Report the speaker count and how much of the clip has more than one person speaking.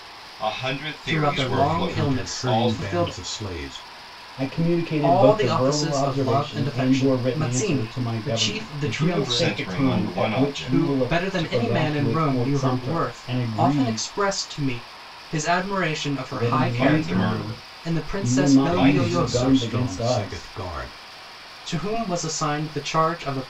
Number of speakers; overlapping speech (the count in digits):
4, about 64%